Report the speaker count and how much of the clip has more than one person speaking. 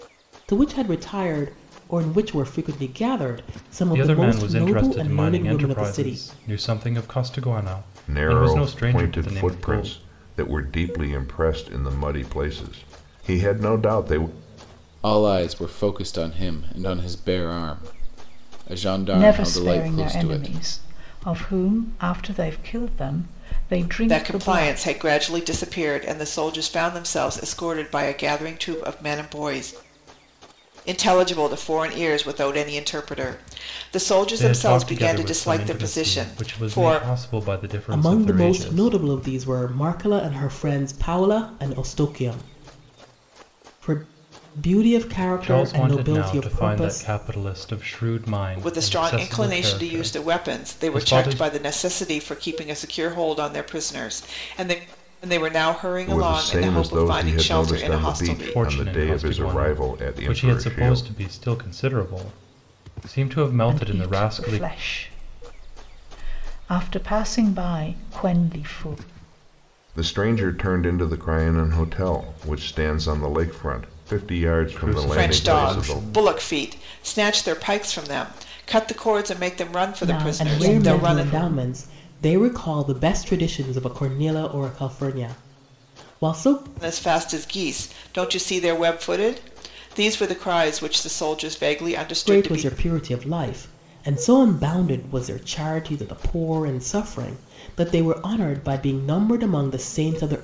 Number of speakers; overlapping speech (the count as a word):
six, about 25%